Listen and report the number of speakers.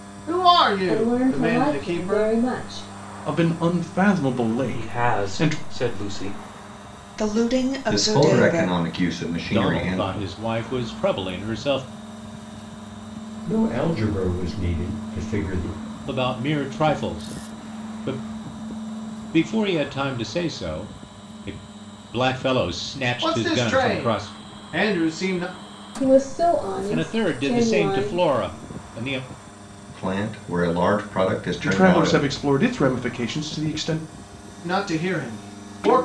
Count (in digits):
8